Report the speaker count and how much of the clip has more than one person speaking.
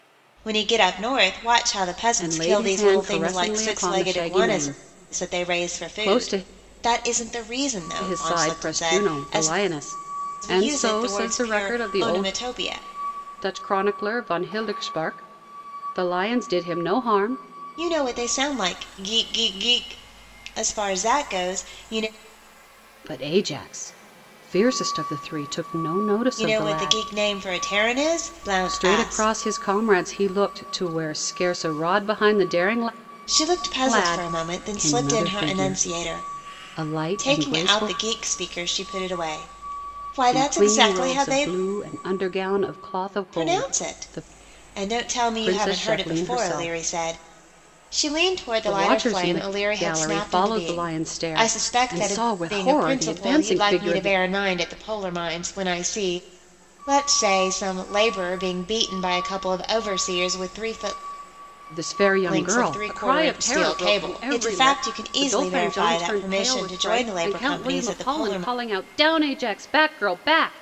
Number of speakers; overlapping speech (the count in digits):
2, about 40%